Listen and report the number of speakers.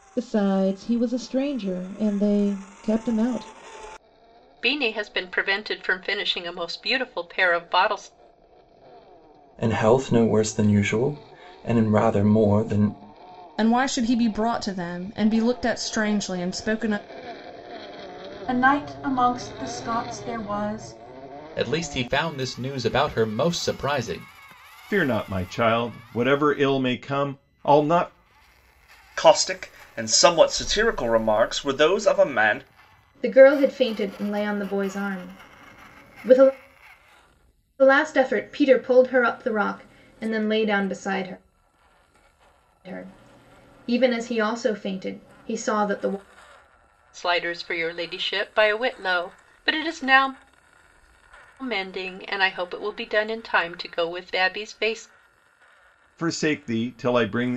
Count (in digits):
9